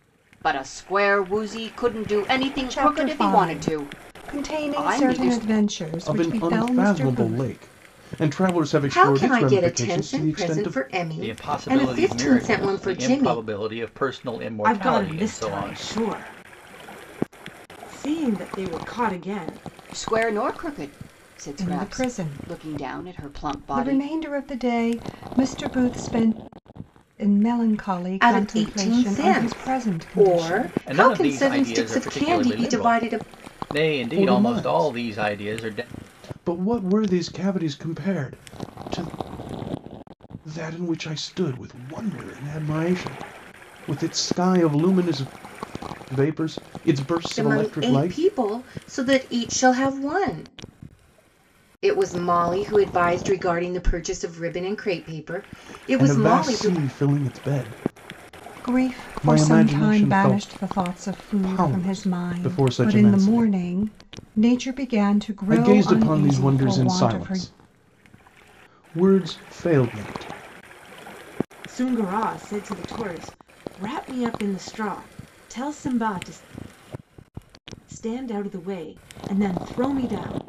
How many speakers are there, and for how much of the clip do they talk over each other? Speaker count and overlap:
6, about 33%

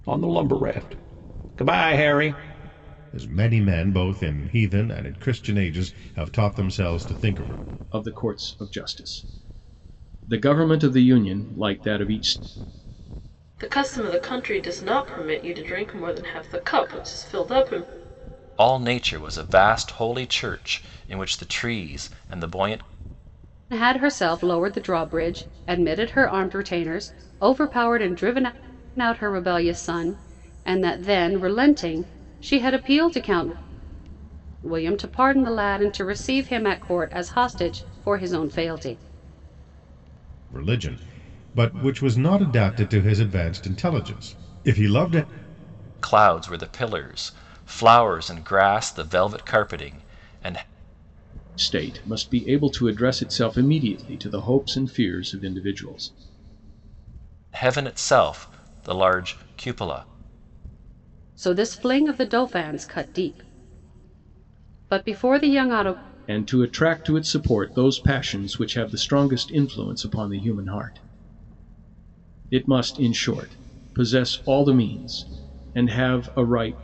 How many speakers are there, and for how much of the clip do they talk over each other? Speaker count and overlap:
6, no overlap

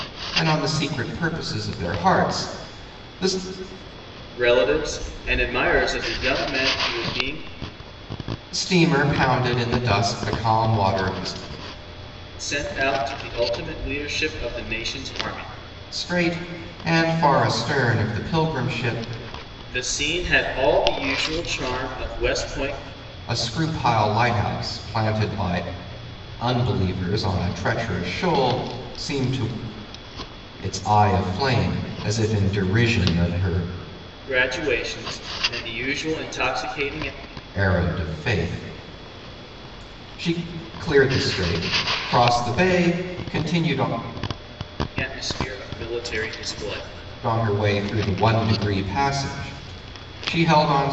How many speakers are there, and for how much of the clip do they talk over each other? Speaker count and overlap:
2, no overlap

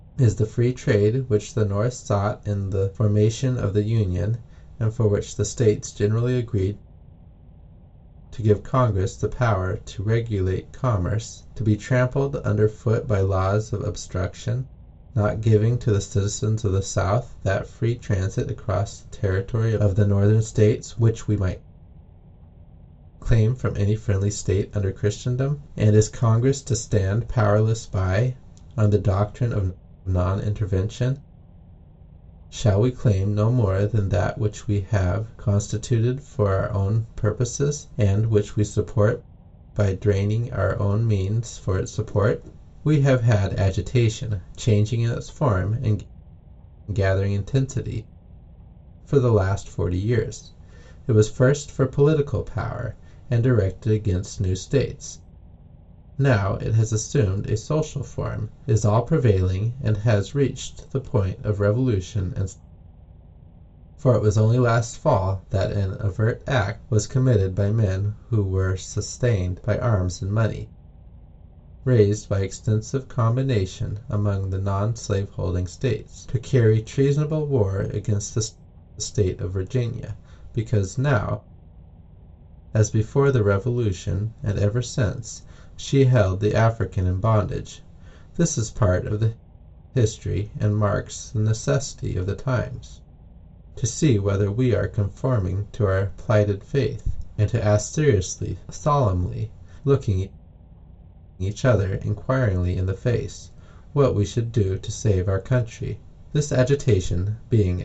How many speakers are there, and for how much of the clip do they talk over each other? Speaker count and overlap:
1, no overlap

